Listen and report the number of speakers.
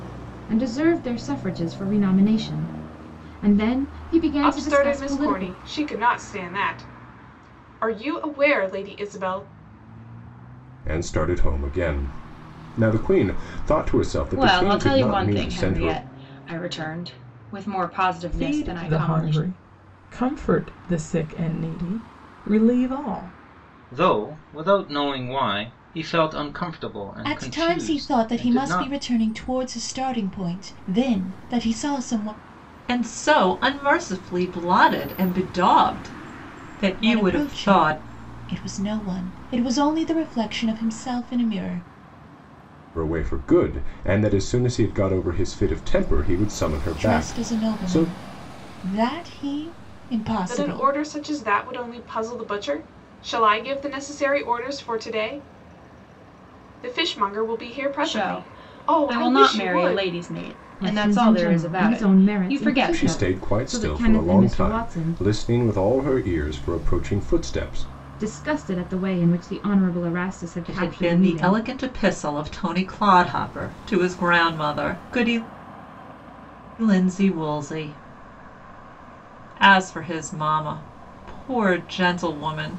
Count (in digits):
8